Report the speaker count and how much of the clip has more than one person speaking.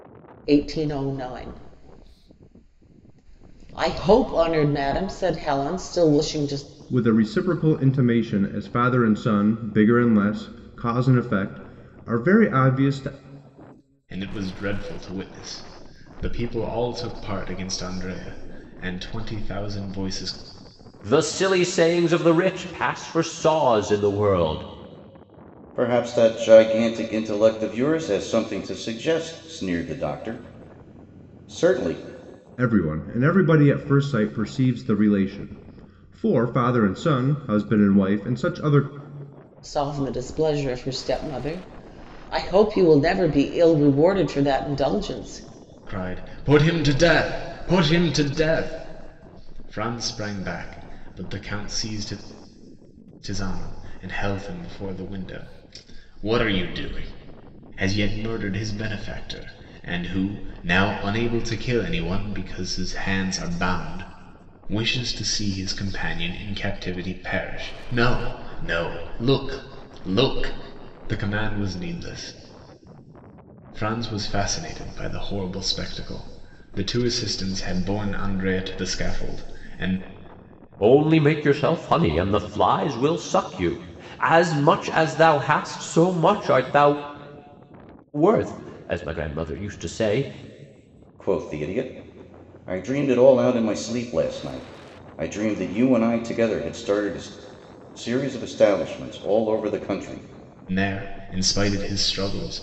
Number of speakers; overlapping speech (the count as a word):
five, no overlap